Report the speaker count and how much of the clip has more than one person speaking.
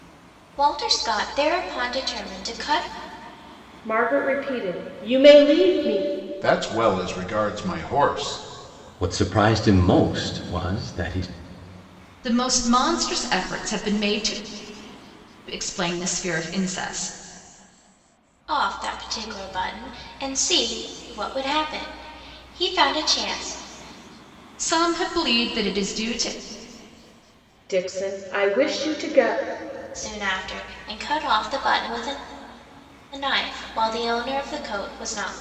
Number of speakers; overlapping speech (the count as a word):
five, no overlap